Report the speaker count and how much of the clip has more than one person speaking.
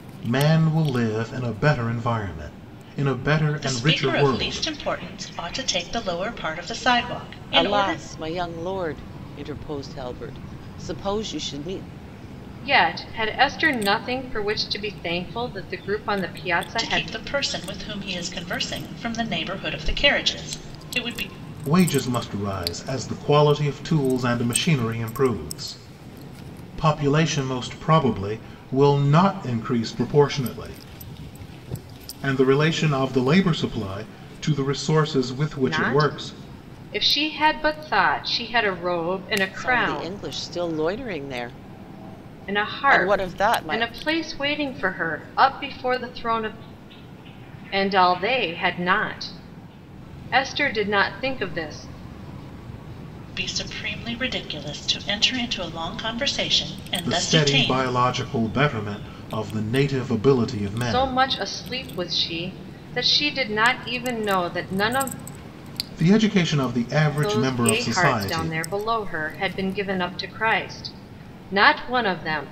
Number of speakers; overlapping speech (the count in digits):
4, about 10%